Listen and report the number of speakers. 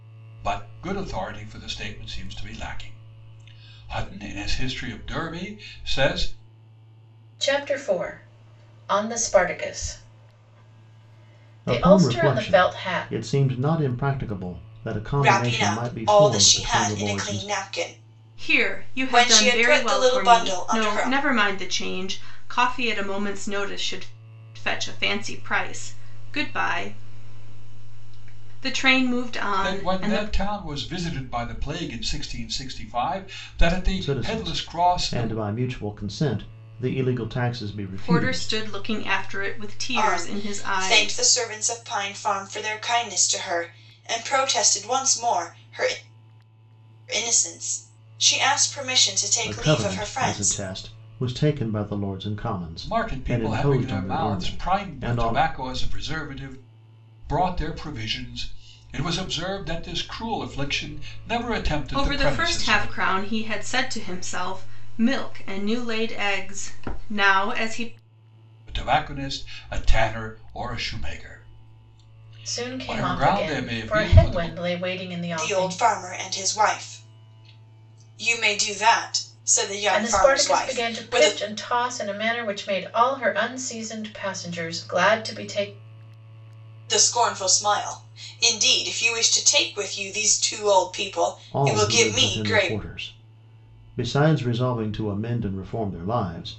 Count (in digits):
5